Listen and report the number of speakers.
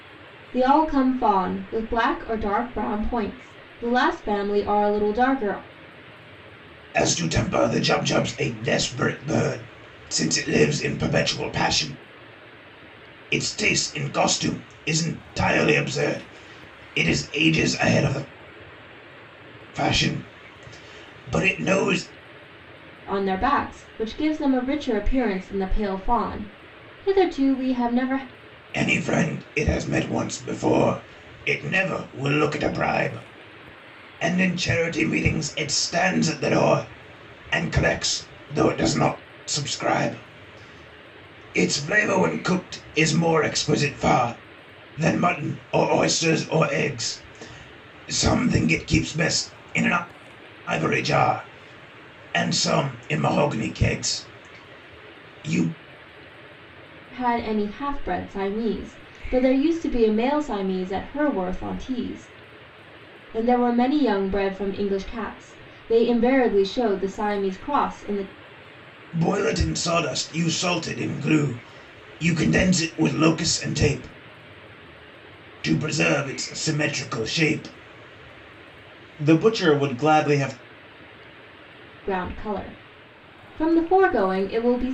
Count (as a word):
two